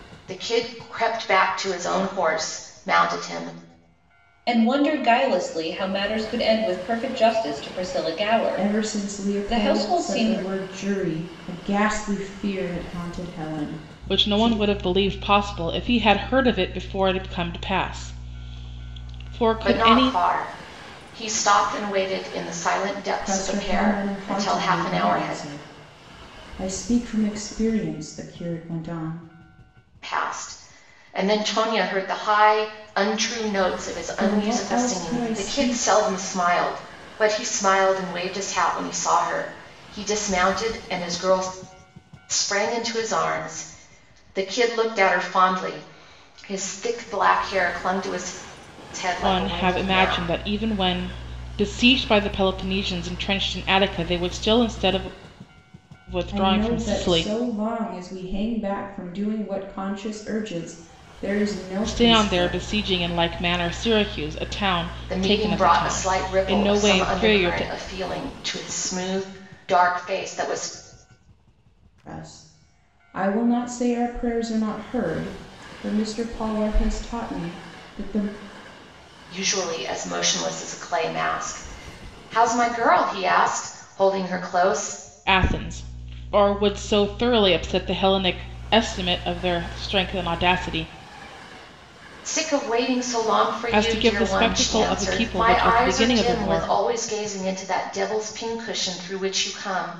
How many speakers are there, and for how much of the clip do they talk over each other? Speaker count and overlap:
4, about 16%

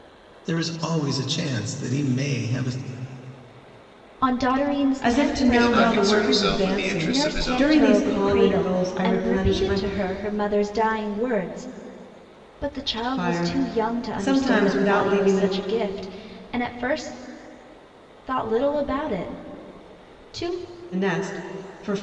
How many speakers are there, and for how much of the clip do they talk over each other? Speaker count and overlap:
4, about 33%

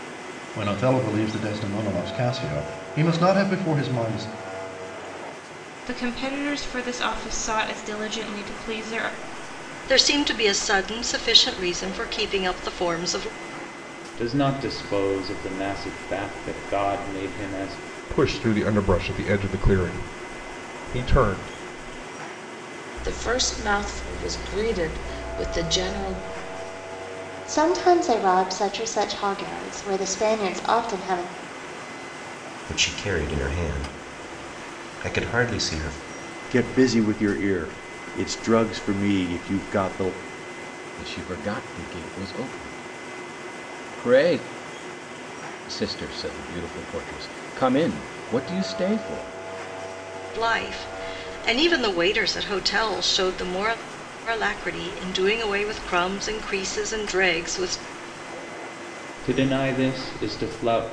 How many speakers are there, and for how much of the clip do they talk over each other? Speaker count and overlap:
10, no overlap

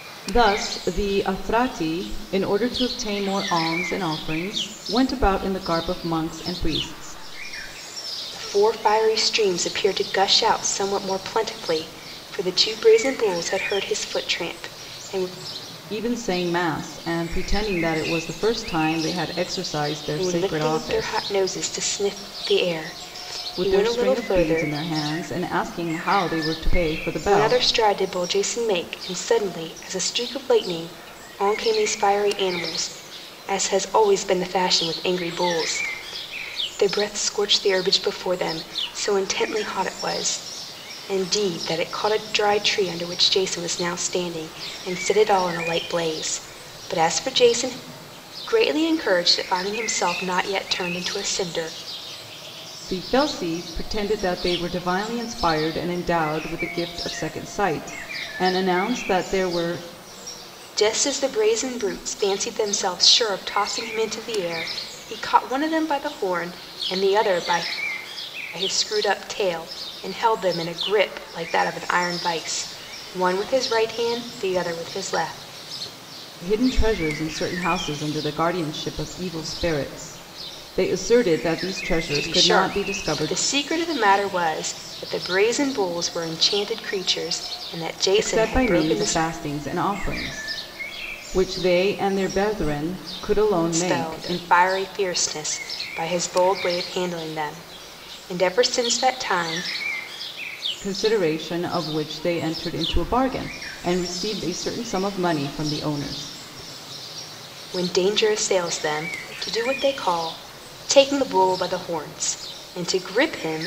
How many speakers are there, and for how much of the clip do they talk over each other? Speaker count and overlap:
2, about 5%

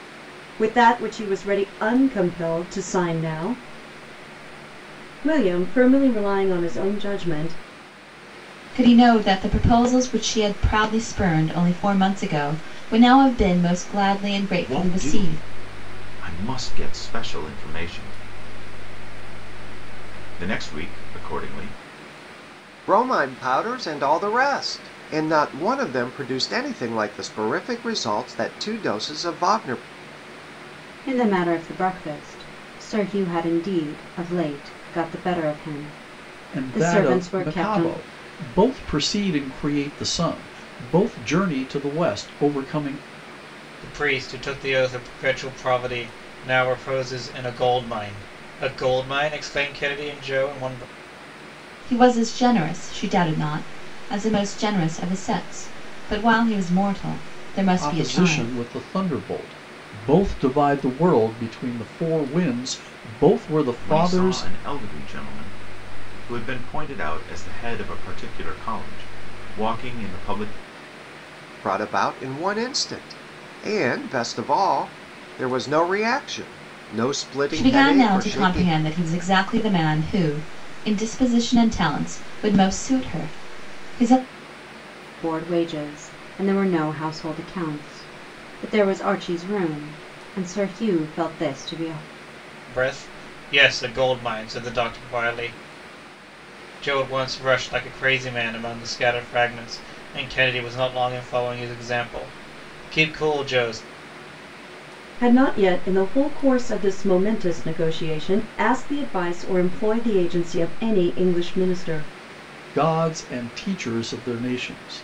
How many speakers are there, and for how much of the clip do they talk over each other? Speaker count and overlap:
7, about 5%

